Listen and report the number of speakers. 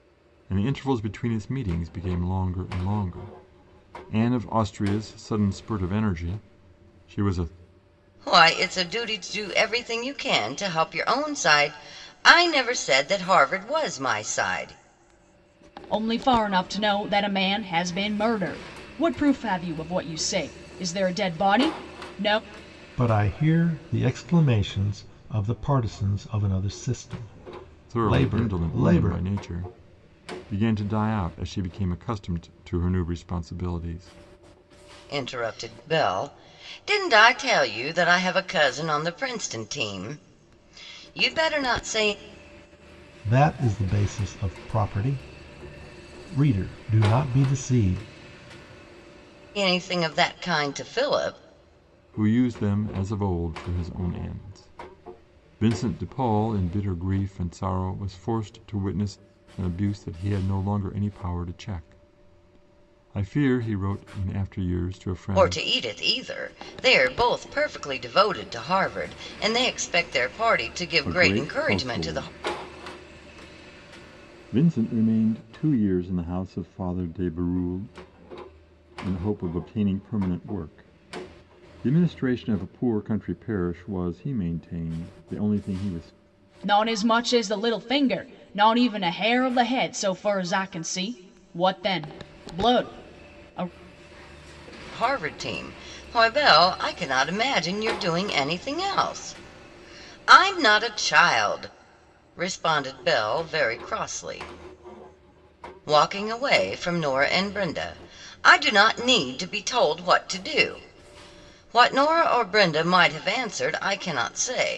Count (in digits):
4